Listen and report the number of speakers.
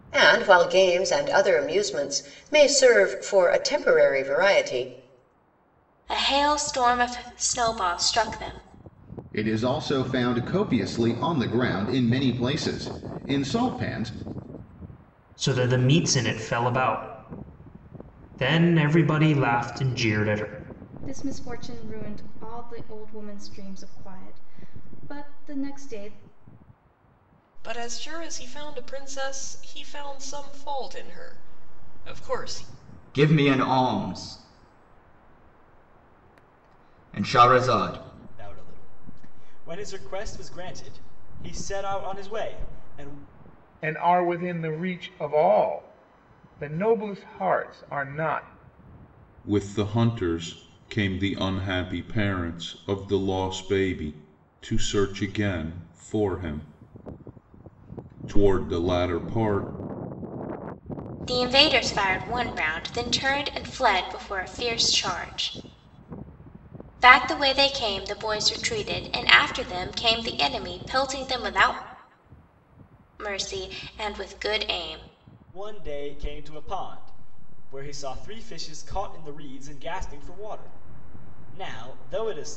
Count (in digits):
10